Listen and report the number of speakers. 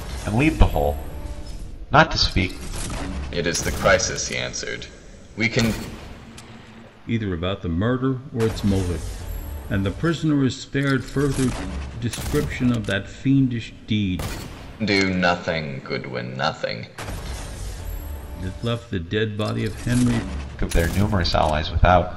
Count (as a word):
three